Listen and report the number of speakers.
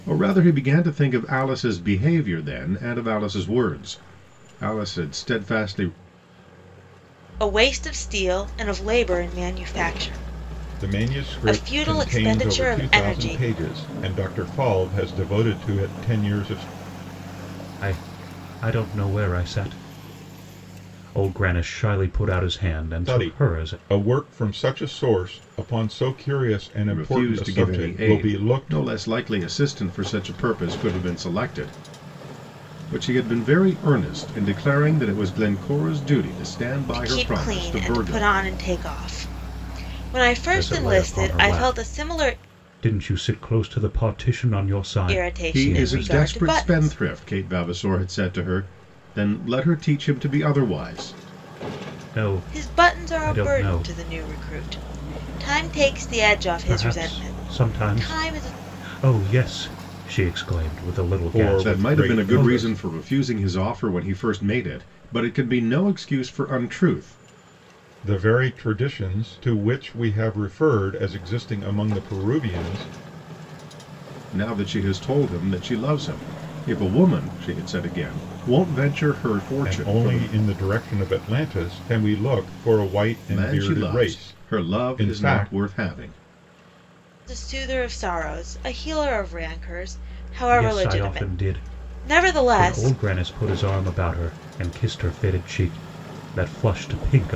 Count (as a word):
four